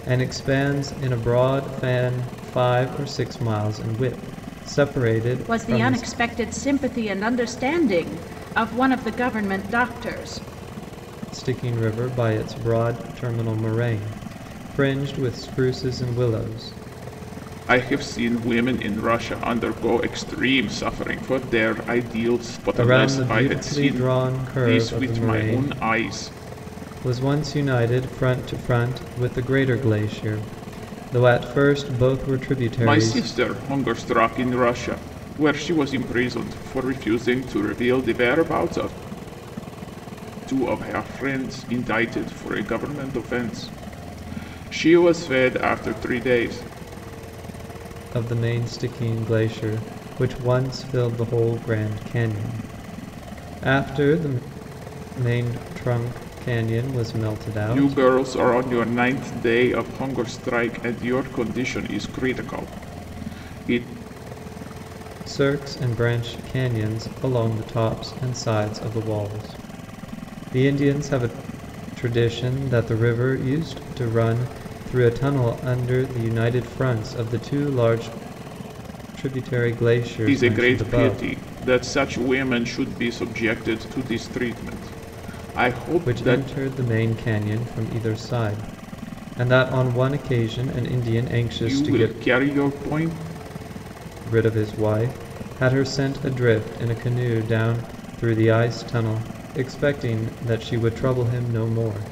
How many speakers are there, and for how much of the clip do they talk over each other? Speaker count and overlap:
2, about 6%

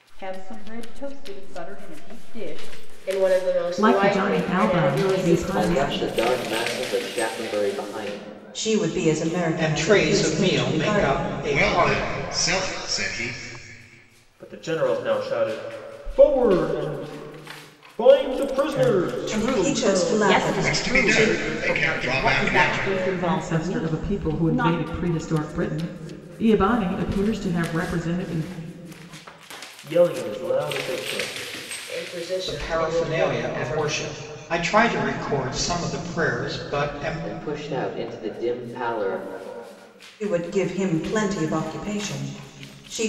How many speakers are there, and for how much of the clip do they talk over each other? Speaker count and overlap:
9, about 30%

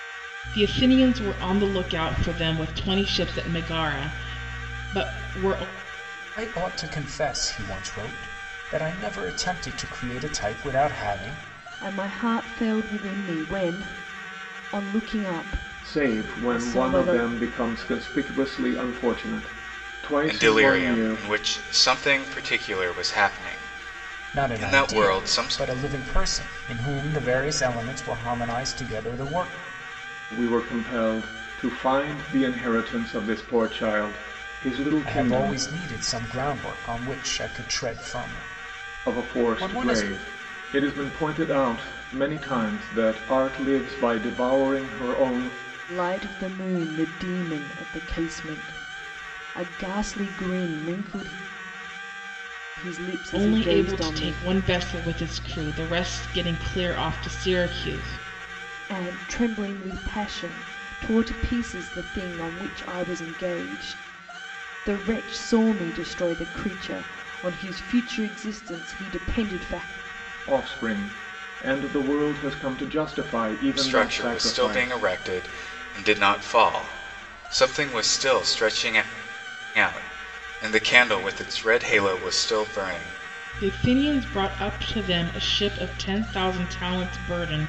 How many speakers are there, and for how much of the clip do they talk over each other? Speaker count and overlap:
5, about 9%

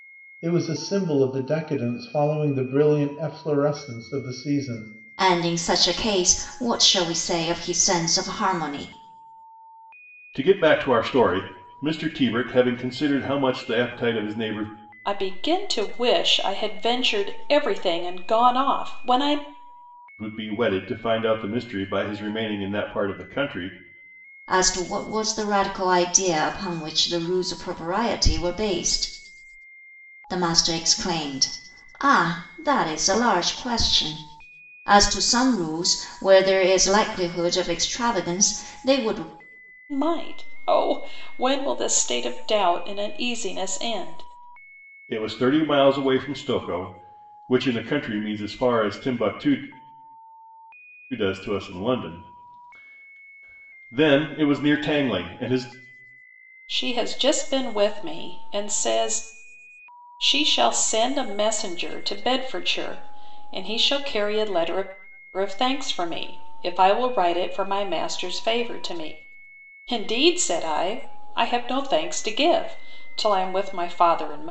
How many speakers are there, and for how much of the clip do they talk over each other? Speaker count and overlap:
4, no overlap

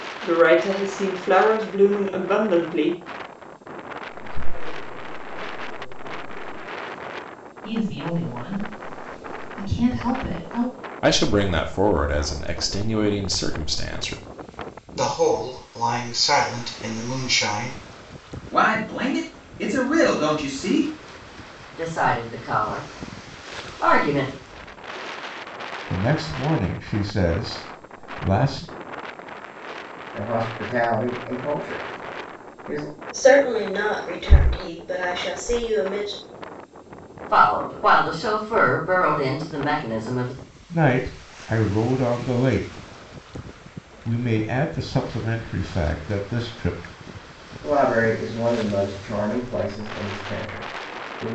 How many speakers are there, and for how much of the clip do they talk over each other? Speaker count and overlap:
10, no overlap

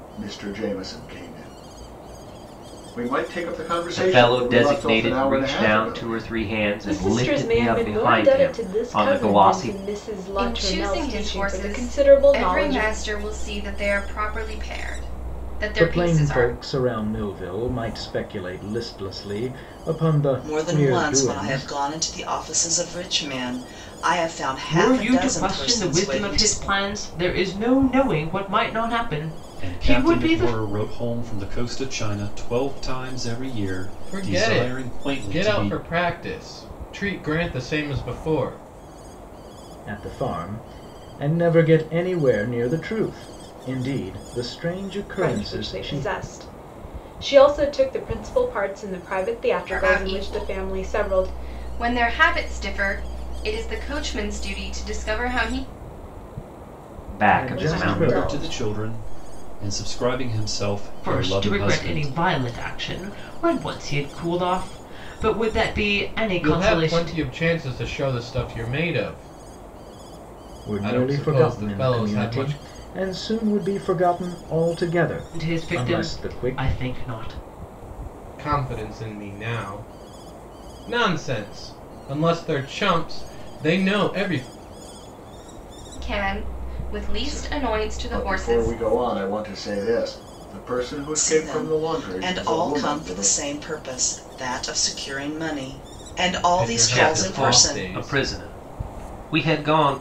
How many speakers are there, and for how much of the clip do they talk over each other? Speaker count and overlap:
9, about 29%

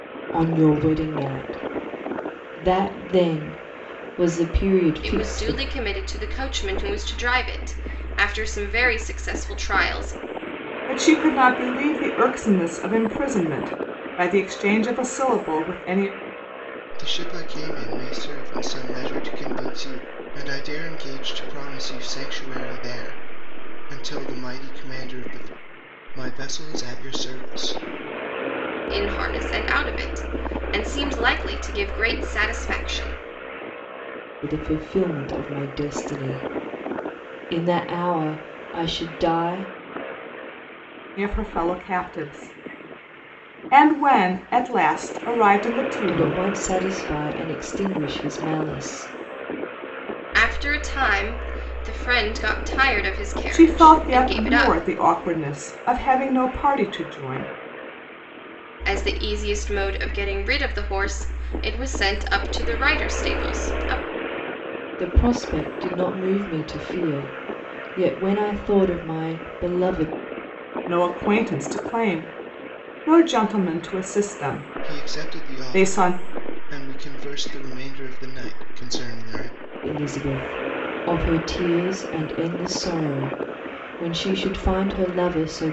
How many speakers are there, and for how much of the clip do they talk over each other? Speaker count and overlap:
4, about 4%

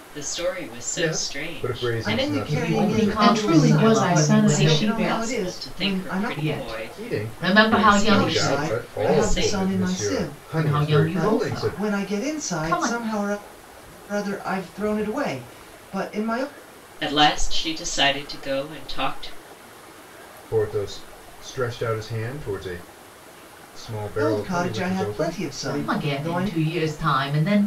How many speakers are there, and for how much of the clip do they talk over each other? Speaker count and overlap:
5, about 51%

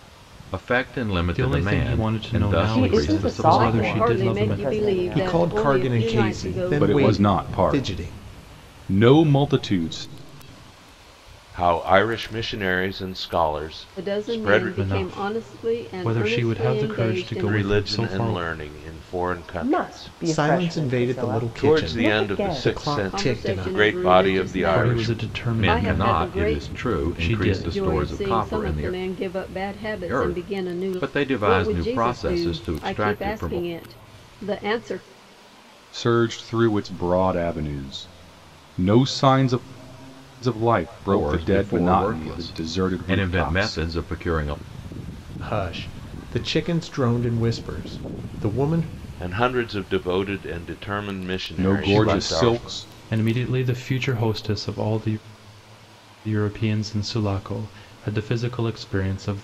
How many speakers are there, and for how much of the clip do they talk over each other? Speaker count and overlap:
7, about 47%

